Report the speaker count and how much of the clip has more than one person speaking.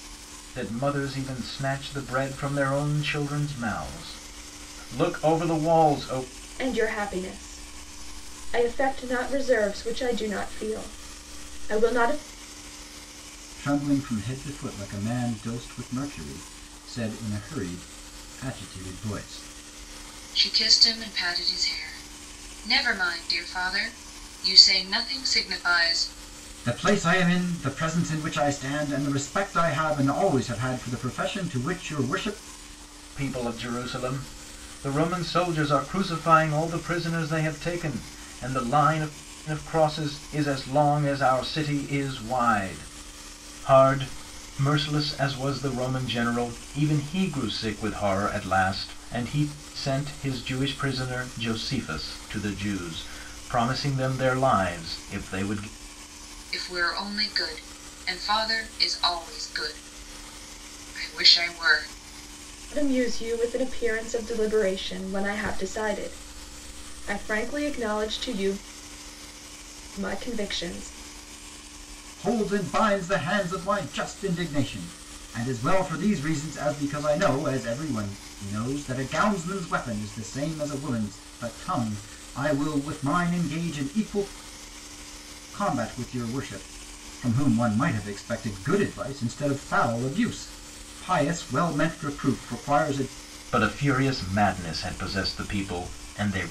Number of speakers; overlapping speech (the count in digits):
4, no overlap